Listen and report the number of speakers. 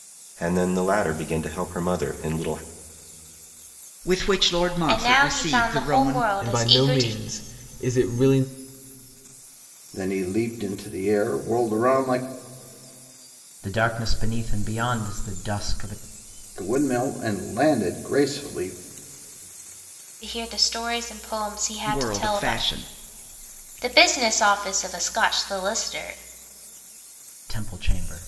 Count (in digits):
6